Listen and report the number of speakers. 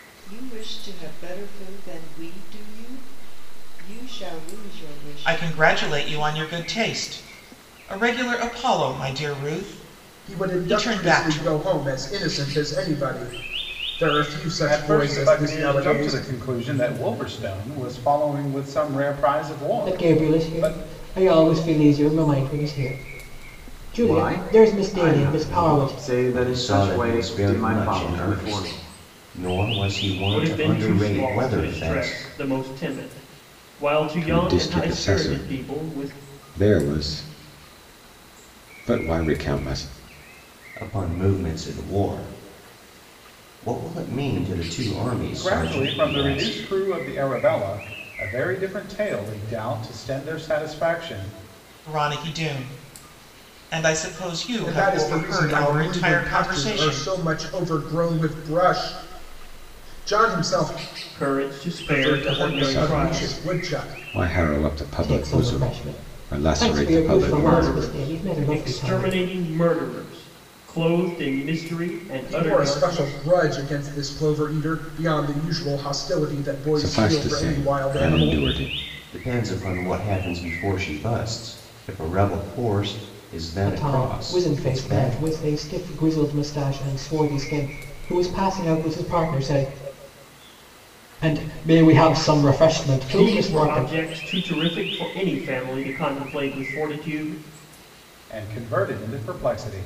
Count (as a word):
nine